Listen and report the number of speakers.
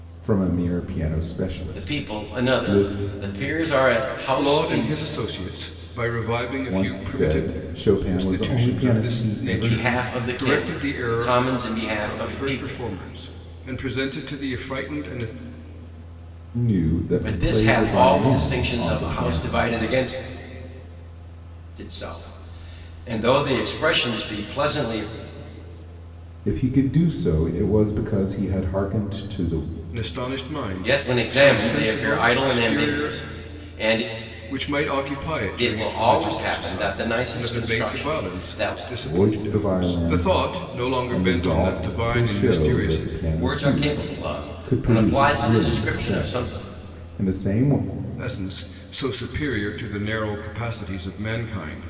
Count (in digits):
3